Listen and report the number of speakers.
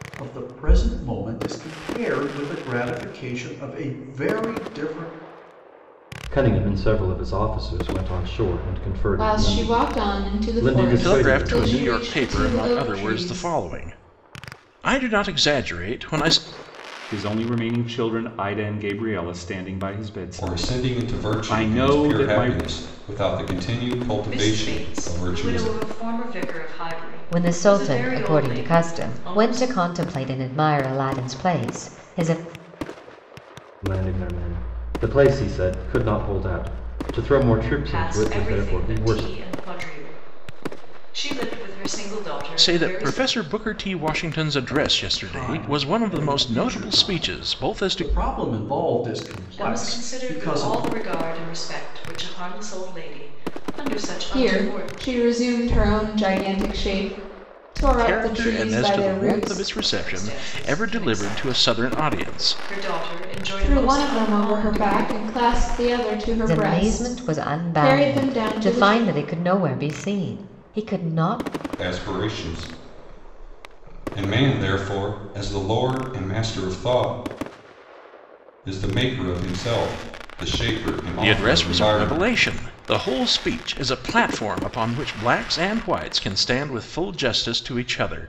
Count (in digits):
8